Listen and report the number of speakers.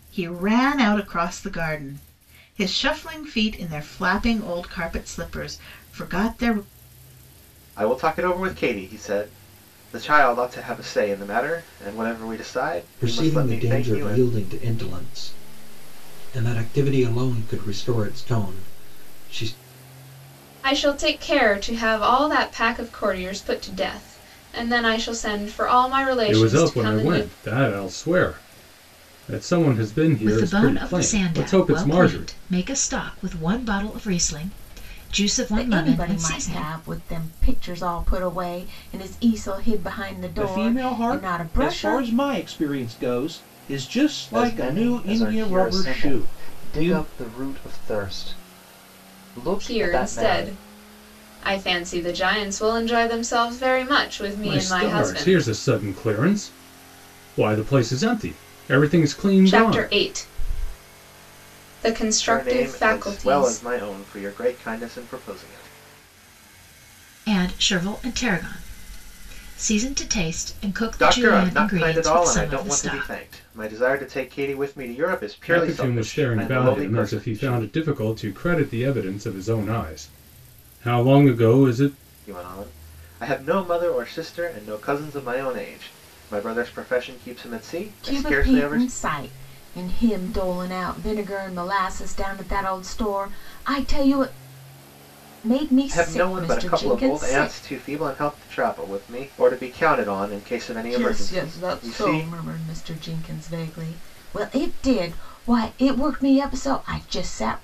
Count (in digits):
9